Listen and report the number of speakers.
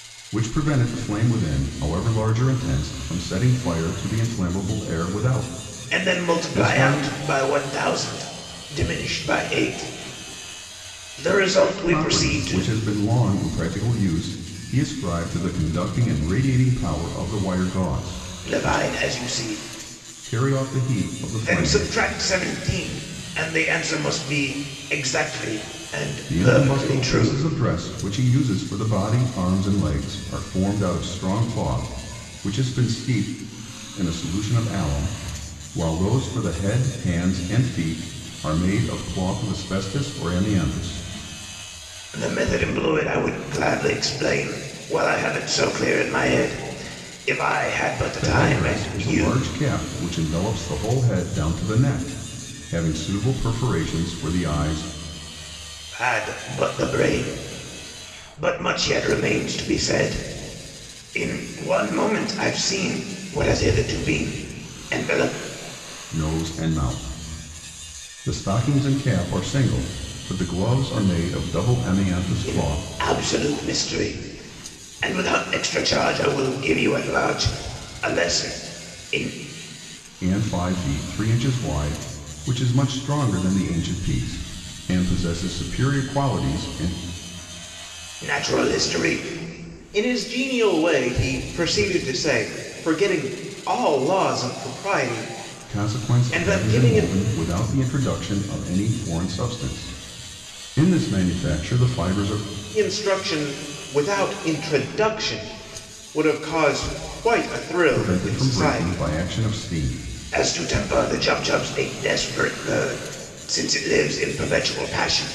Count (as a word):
two